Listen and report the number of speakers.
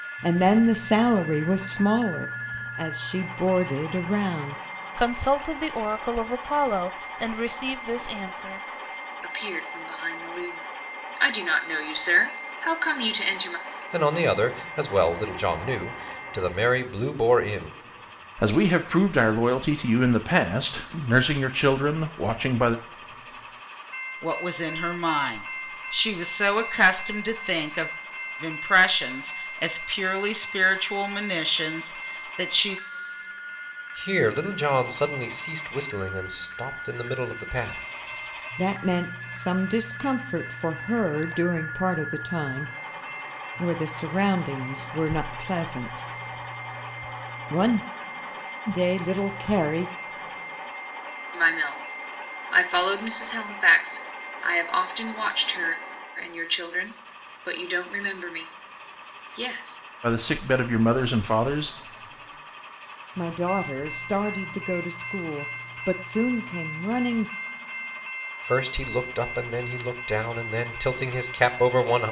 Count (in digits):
6